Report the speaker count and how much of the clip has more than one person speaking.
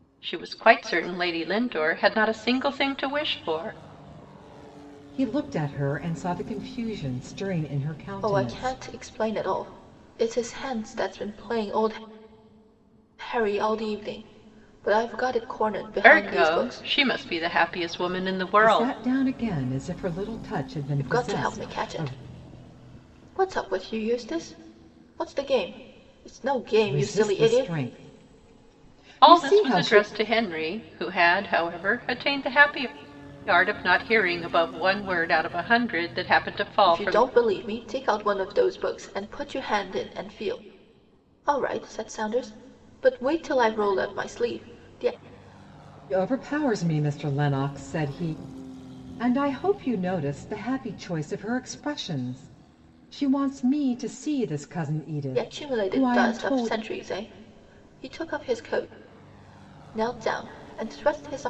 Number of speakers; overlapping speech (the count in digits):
3, about 11%